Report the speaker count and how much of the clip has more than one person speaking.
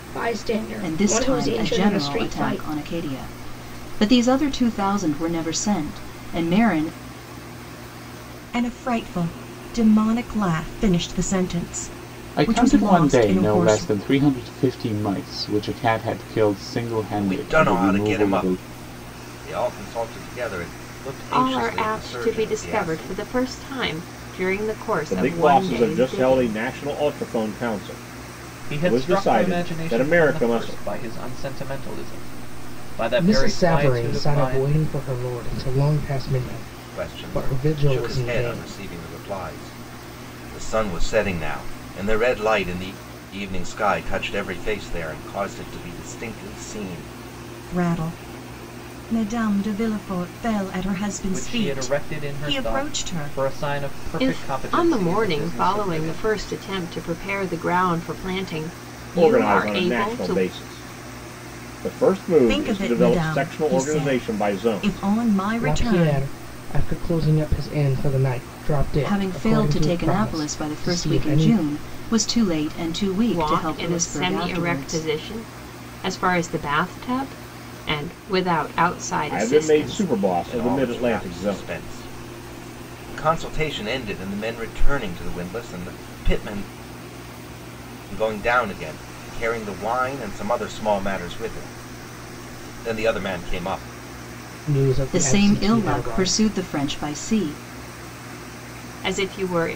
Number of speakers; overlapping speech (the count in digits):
8, about 31%